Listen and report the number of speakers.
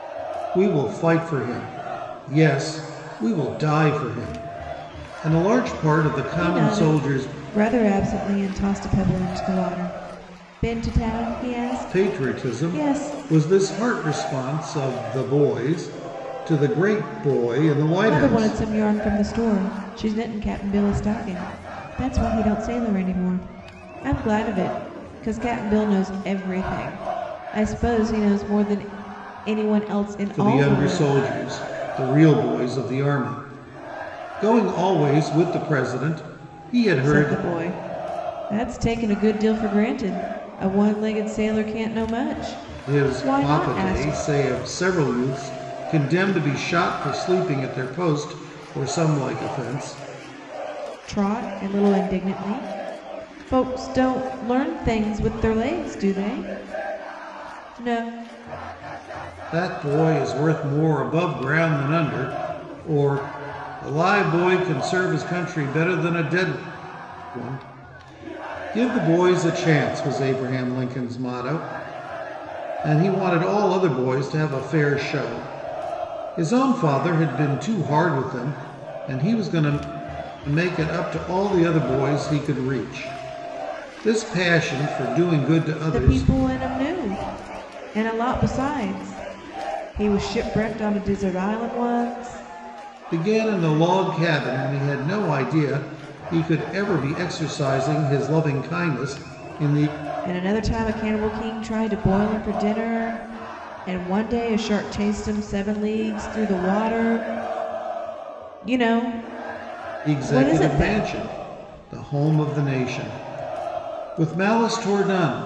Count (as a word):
two